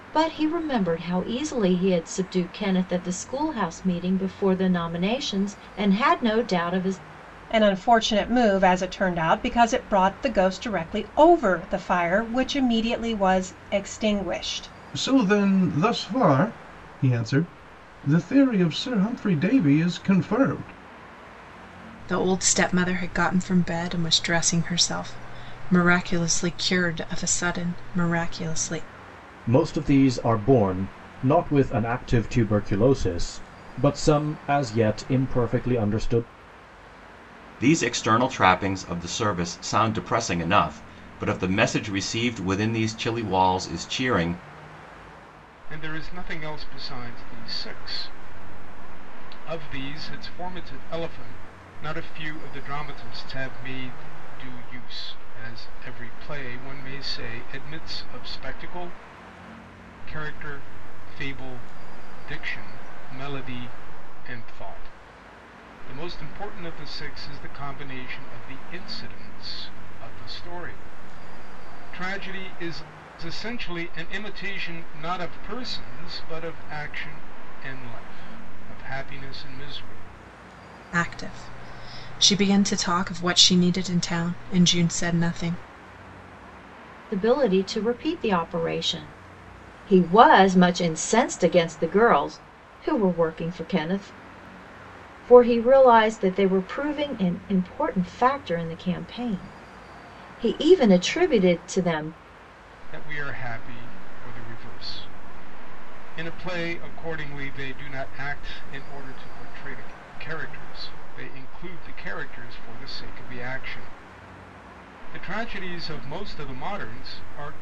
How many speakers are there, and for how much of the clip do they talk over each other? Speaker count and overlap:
7, no overlap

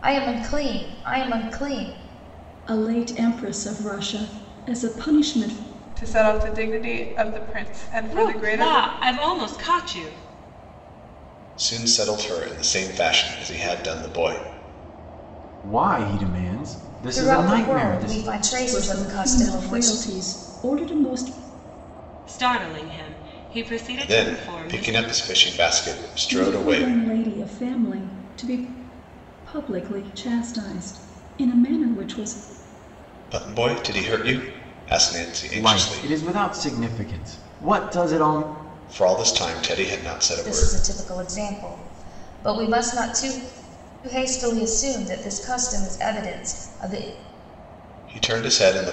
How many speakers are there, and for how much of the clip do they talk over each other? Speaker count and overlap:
6, about 12%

